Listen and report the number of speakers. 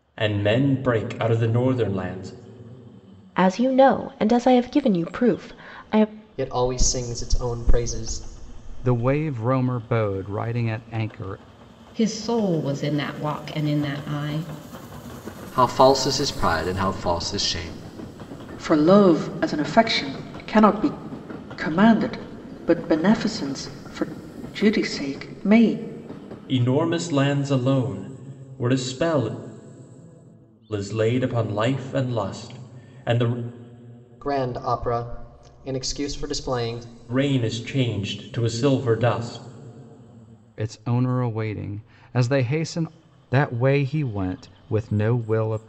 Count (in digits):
7